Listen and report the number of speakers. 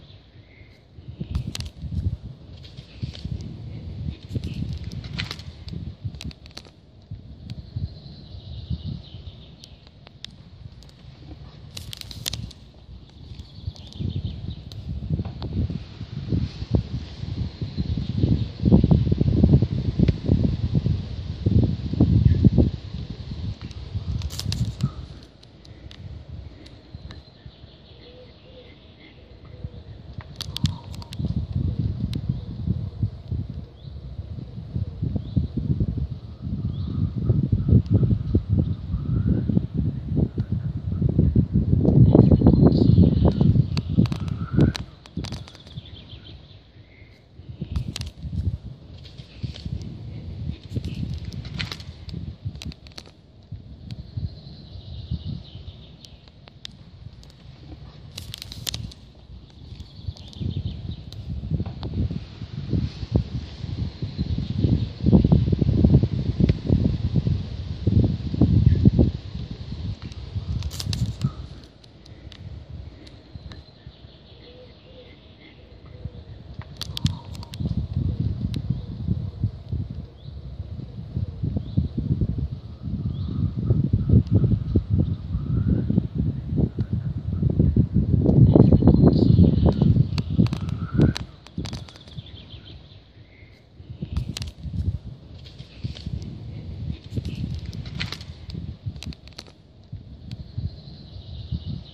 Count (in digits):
0